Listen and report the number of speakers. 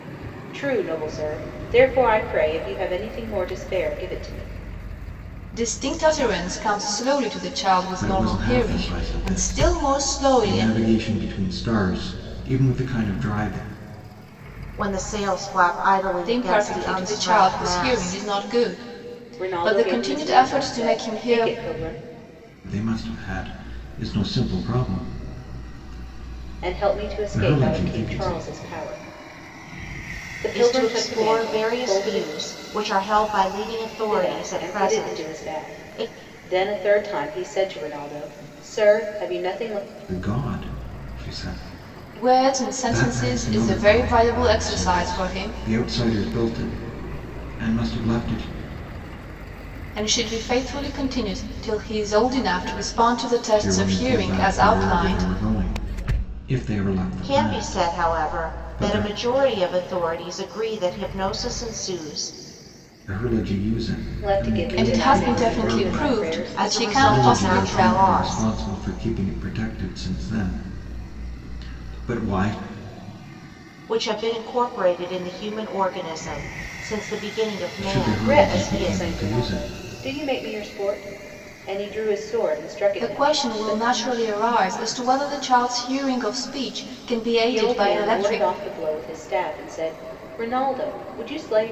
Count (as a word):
four